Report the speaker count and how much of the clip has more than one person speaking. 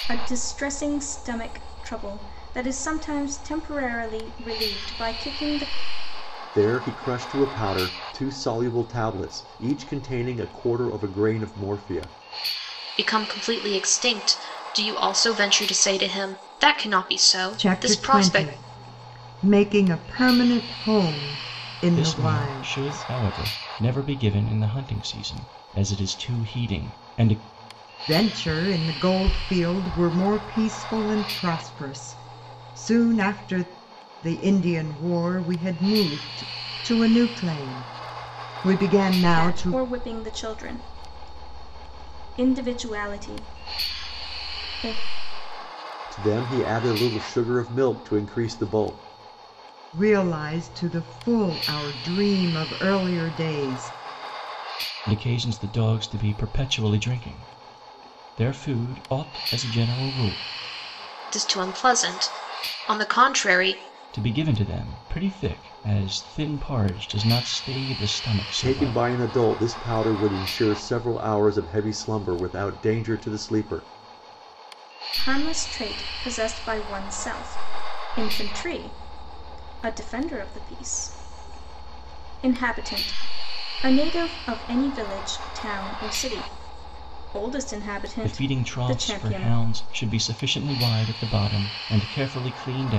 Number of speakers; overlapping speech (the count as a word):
five, about 5%